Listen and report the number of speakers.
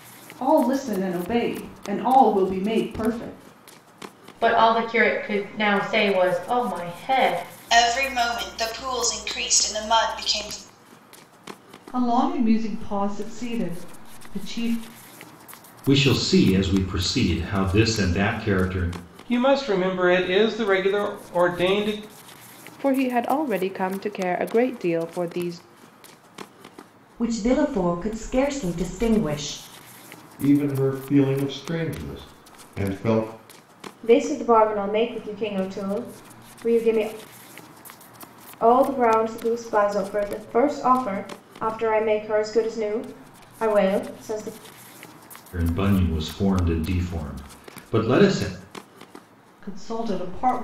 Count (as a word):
ten